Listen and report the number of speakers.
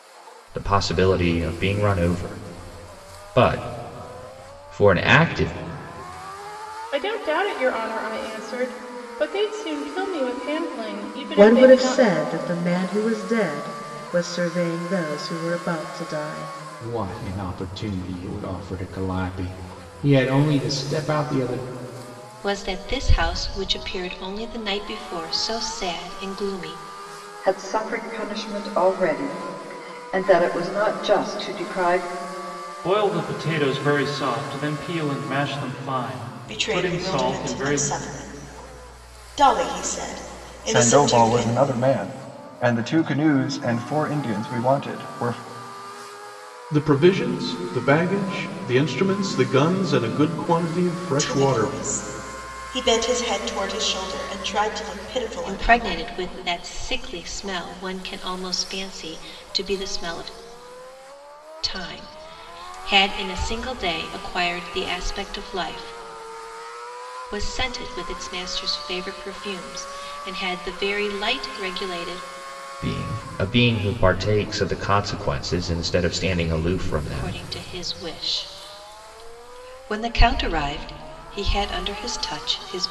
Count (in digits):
10